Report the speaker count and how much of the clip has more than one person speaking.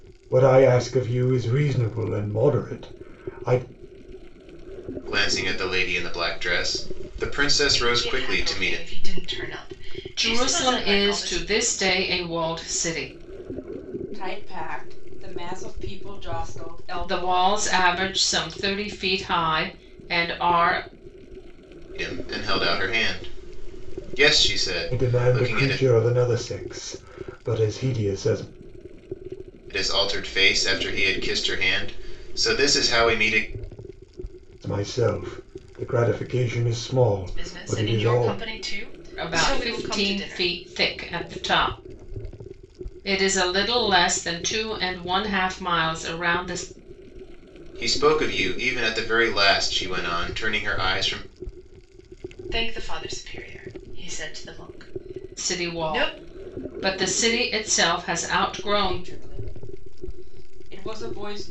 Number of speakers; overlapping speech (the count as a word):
five, about 13%